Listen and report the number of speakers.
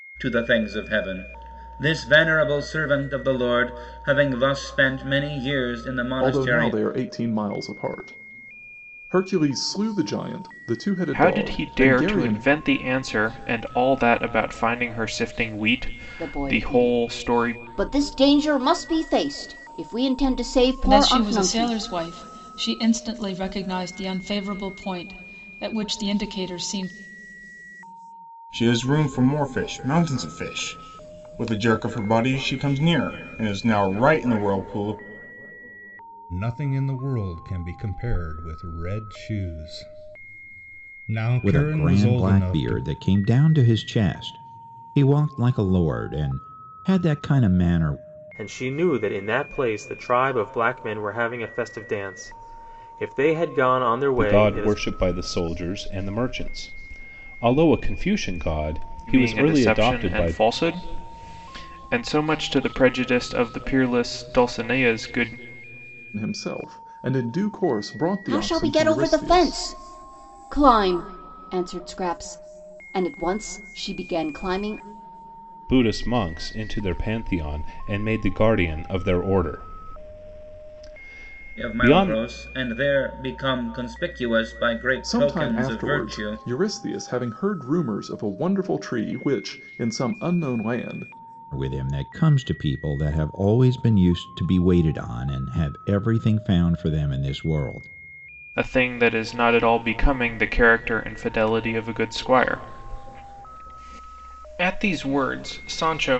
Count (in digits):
10